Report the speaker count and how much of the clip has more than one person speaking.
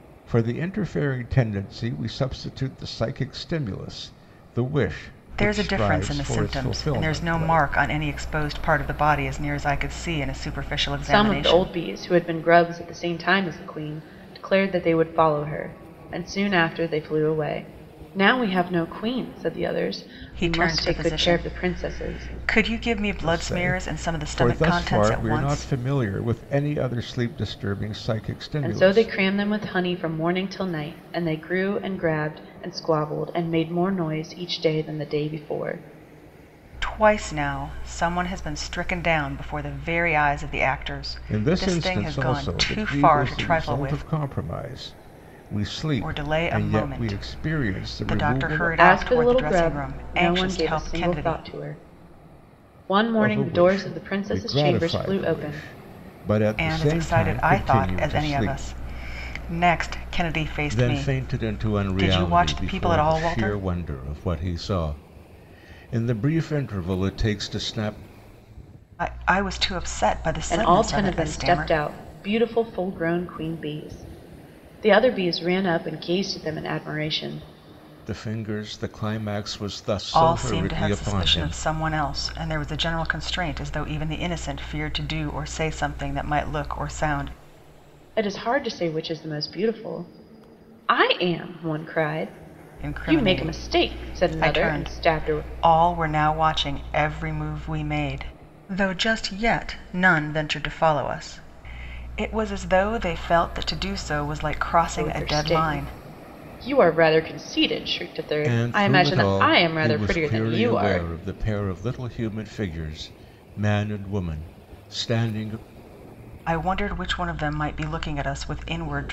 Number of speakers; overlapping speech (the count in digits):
3, about 28%